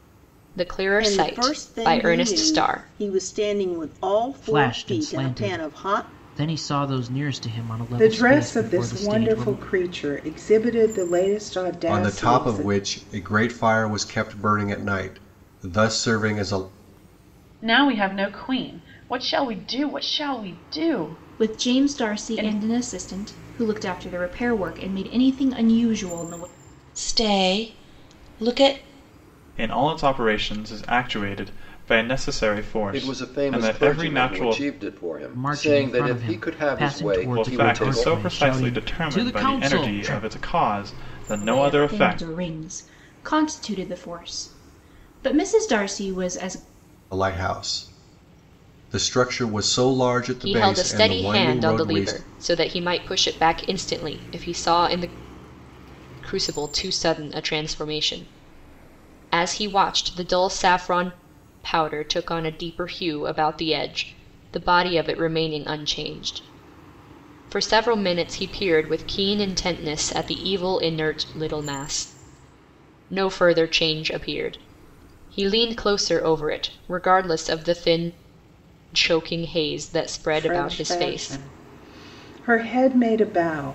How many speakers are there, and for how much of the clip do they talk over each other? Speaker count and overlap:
10, about 22%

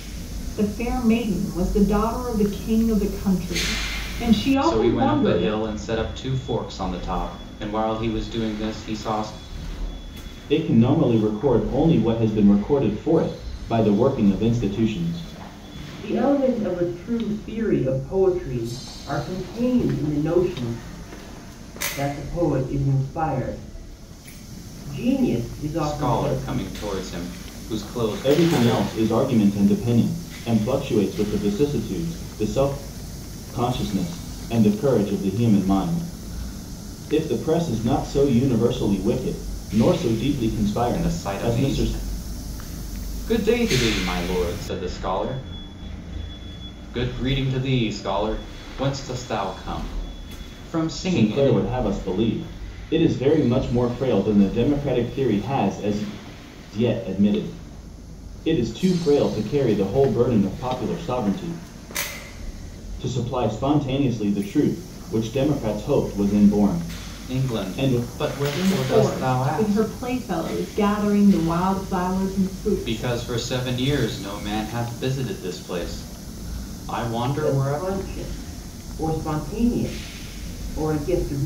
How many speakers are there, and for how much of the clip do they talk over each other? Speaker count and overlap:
4, about 8%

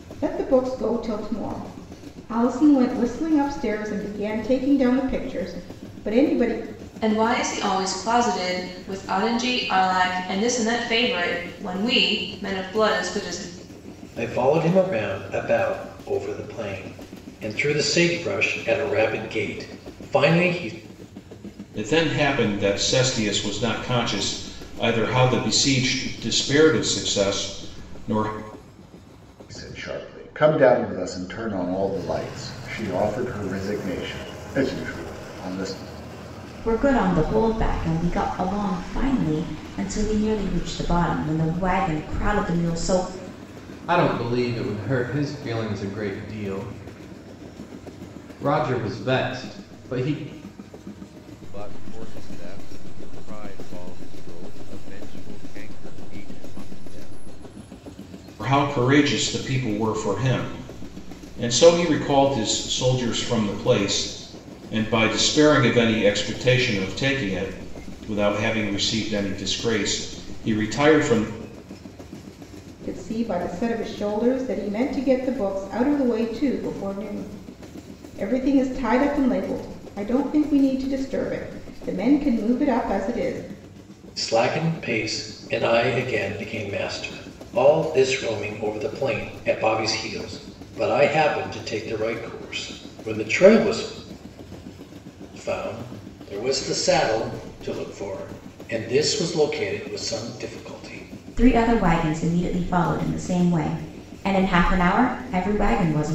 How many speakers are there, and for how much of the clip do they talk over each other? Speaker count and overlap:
8, no overlap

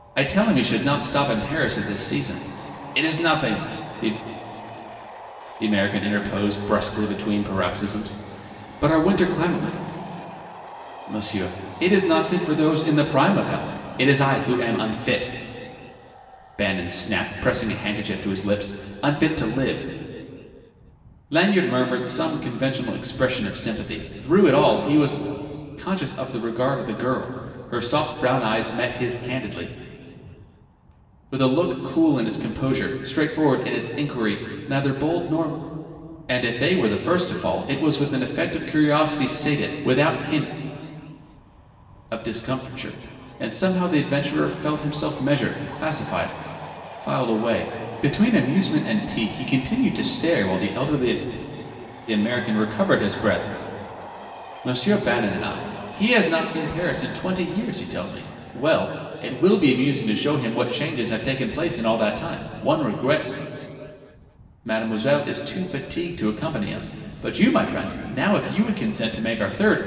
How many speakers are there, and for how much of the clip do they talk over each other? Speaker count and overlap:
1, no overlap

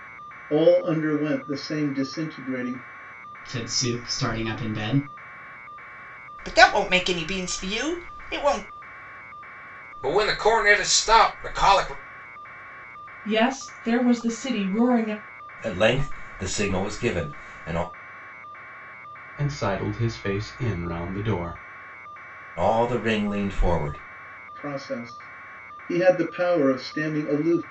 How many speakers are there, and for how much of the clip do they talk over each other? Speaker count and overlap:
7, no overlap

